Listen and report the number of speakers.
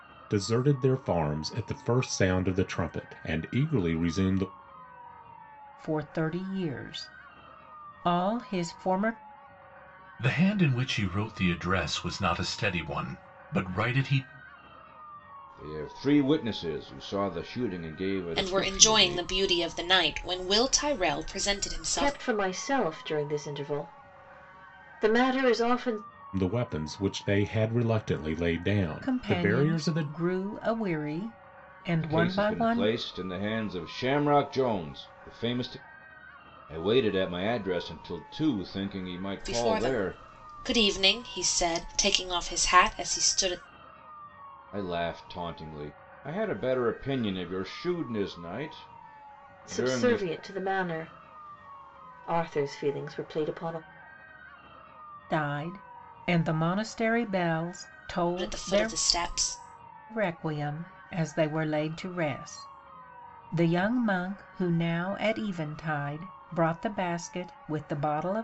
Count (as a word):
six